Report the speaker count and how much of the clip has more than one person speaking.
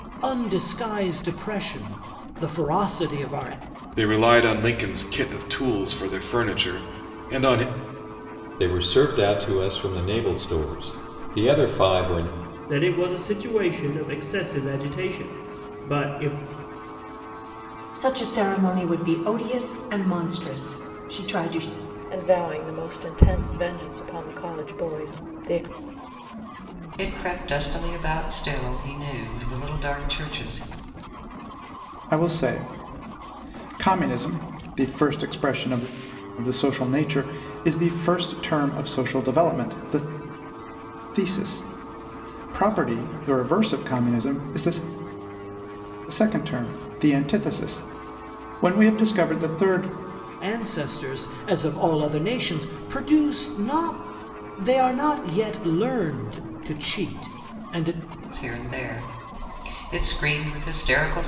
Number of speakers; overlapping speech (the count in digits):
8, no overlap